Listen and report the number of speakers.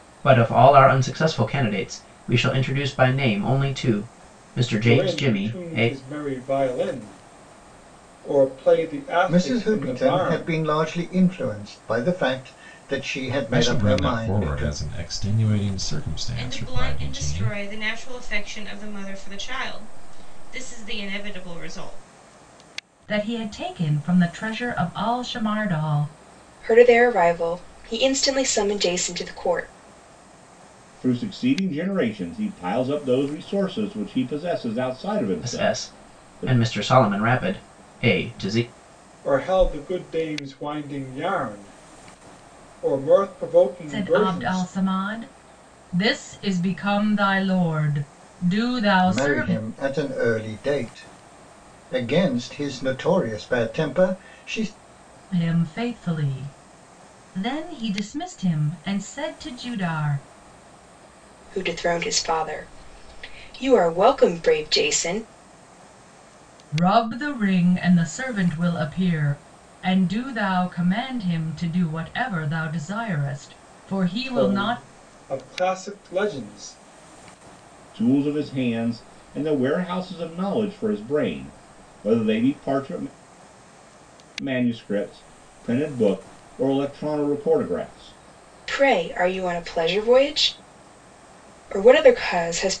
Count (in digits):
8